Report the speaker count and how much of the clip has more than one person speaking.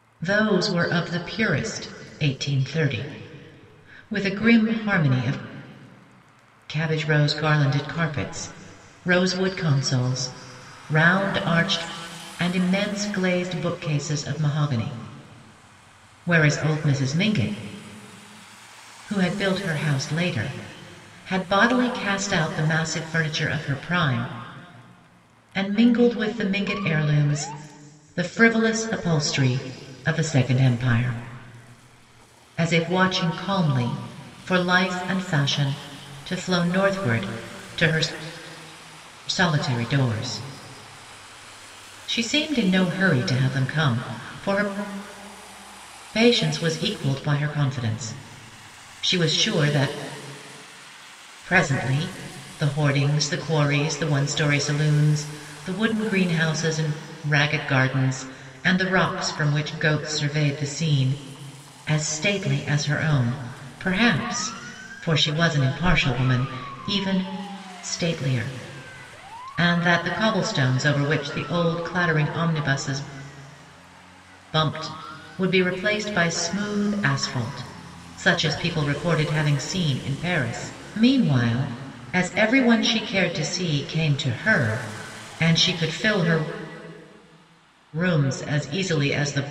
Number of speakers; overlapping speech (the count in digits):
1, no overlap